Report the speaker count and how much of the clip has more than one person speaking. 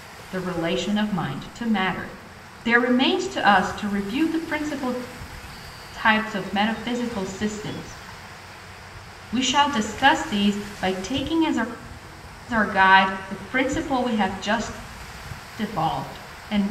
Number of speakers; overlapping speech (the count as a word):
one, no overlap